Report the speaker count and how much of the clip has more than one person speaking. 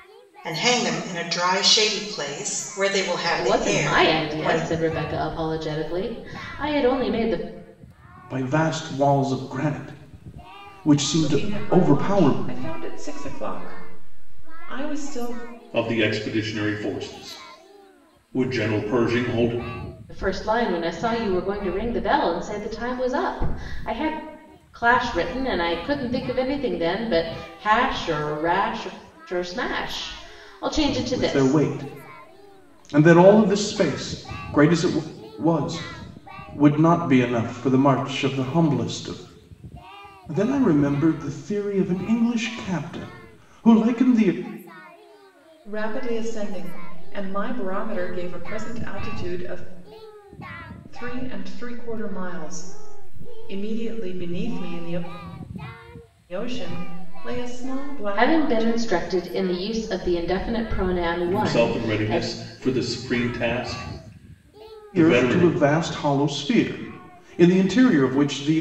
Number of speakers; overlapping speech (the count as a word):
five, about 8%